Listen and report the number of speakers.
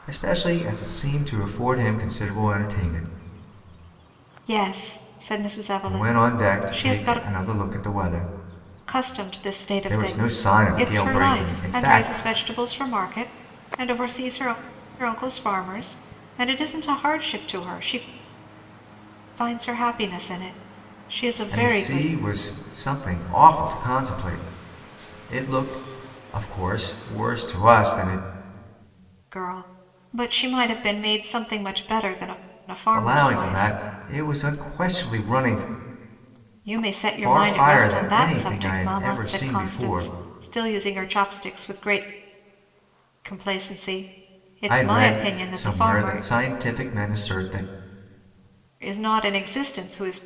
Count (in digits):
2